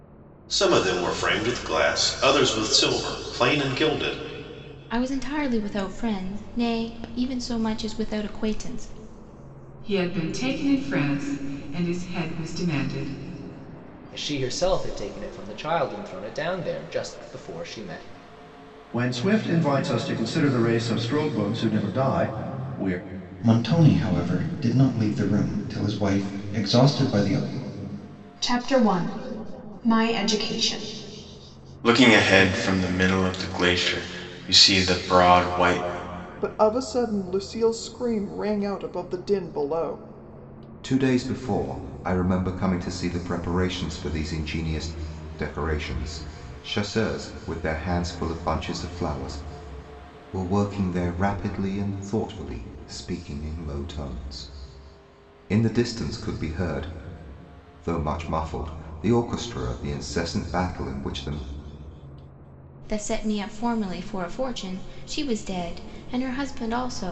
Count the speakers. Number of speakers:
10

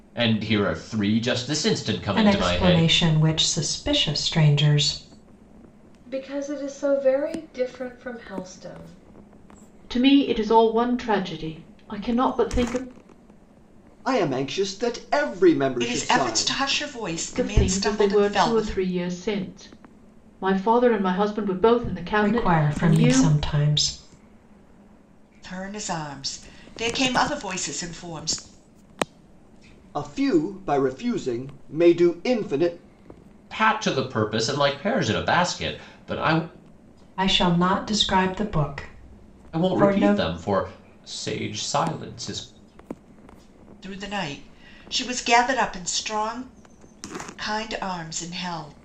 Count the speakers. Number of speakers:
6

